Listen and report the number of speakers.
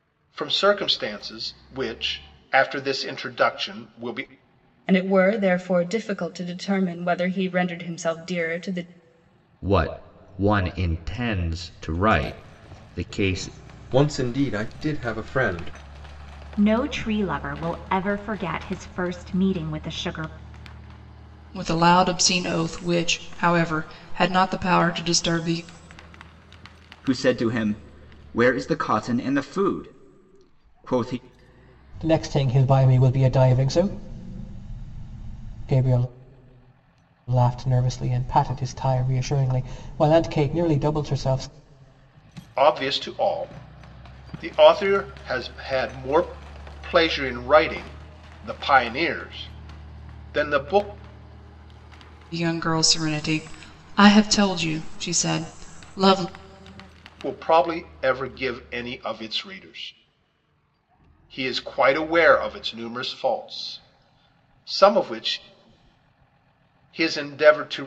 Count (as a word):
eight